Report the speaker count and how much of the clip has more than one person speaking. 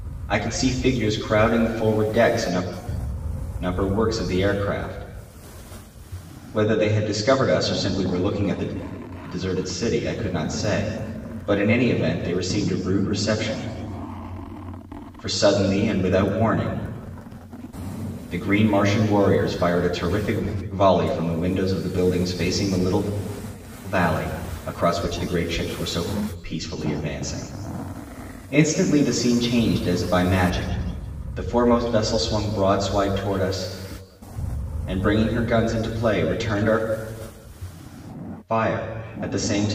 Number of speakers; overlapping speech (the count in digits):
1, no overlap